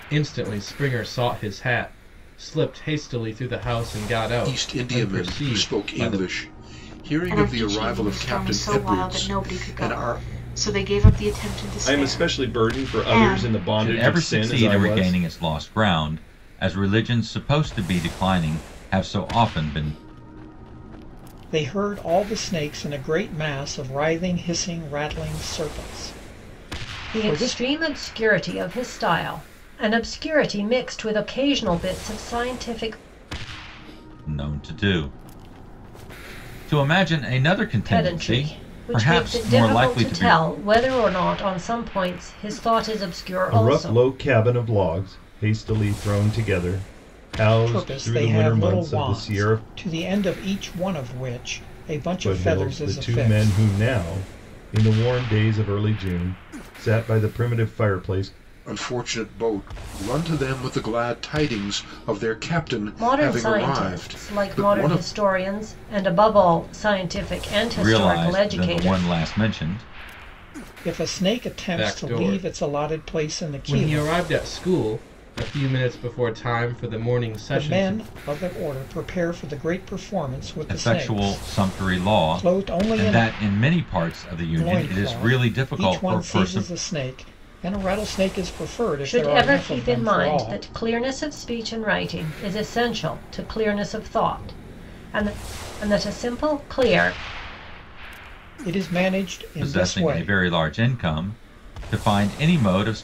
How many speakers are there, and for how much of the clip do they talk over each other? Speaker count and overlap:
7, about 28%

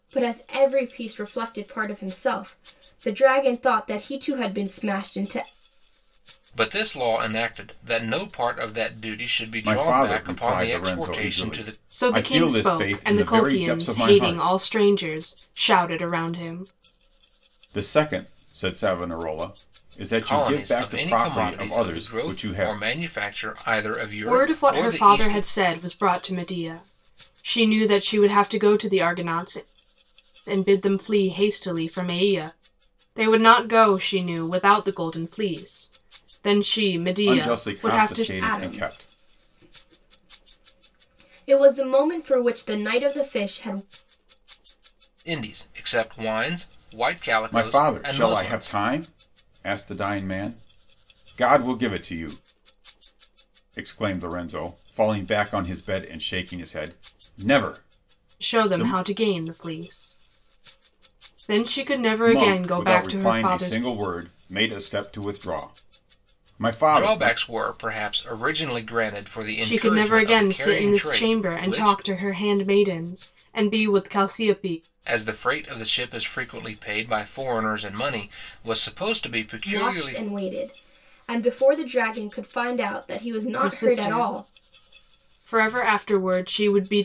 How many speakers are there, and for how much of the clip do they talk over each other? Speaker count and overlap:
4, about 21%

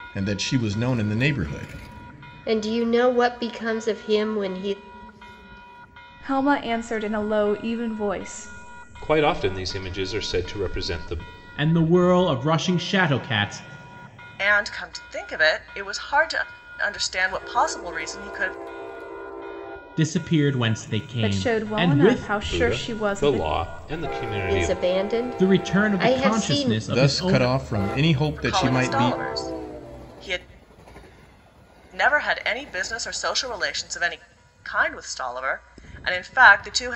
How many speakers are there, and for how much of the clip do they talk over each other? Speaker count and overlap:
6, about 15%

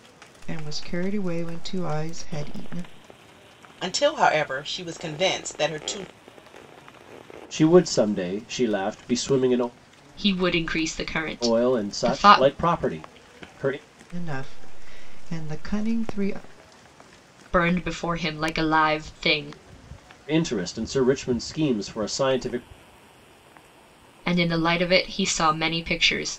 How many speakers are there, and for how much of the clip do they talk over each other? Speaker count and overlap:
4, about 4%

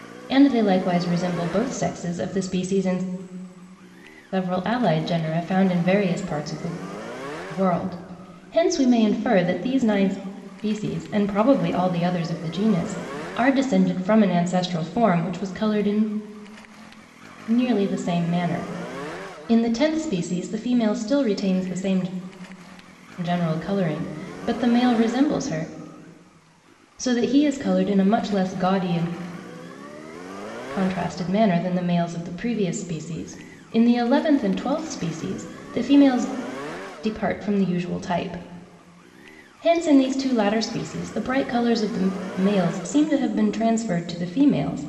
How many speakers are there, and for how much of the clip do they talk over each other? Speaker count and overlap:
1, no overlap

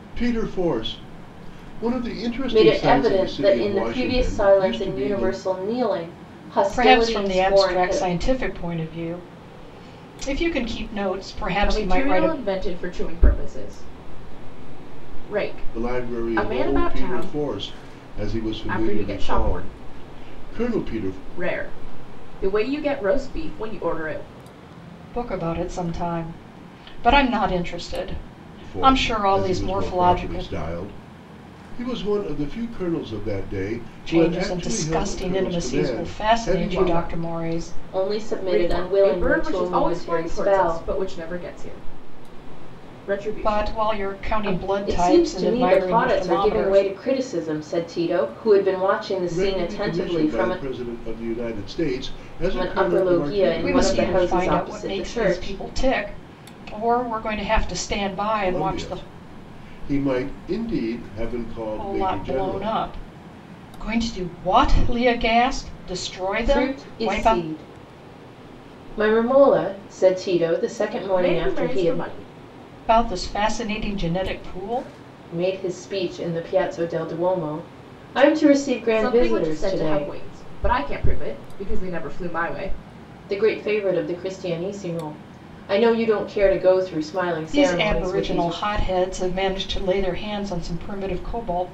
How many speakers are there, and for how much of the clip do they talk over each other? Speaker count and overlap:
4, about 34%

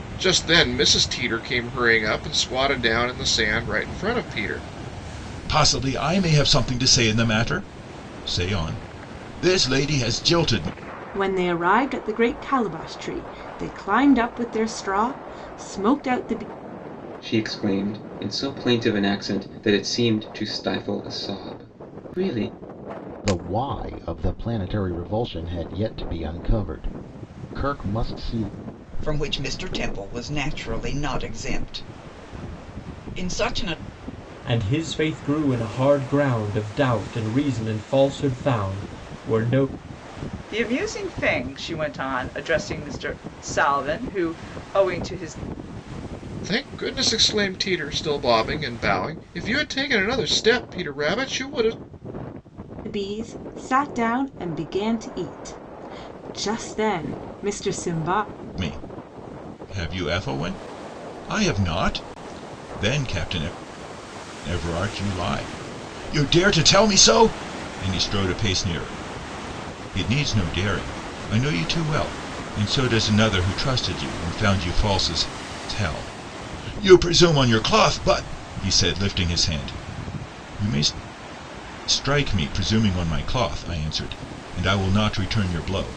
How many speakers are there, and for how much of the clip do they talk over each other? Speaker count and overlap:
8, no overlap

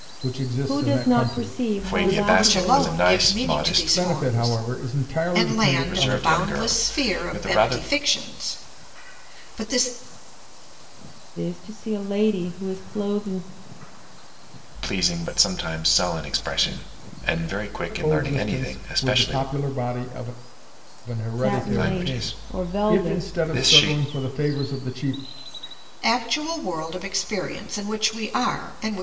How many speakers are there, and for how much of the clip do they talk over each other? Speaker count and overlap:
4, about 37%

